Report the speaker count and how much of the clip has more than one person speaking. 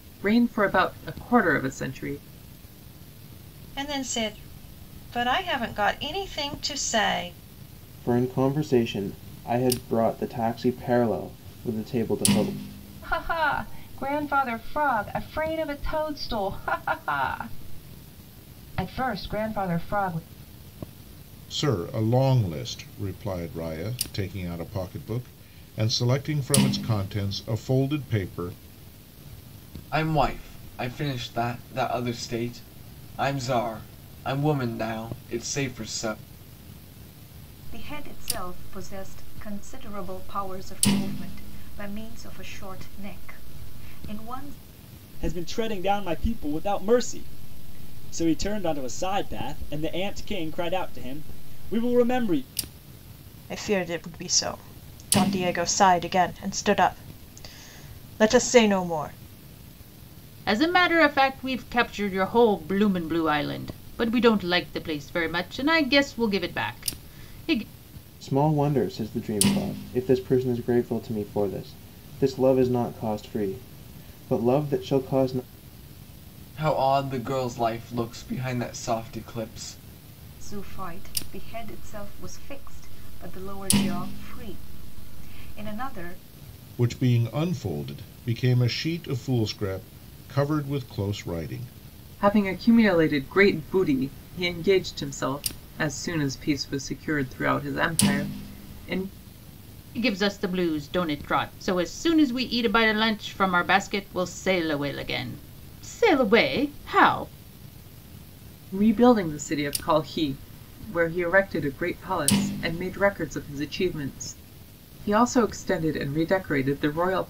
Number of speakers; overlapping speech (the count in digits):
10, no overlap